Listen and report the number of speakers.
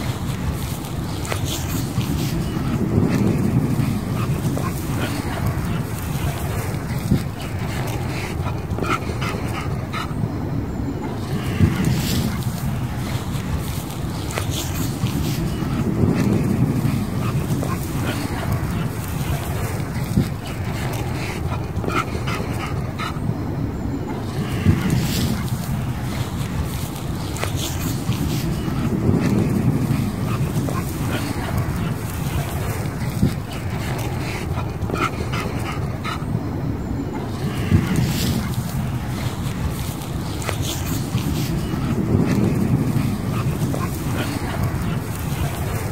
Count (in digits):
0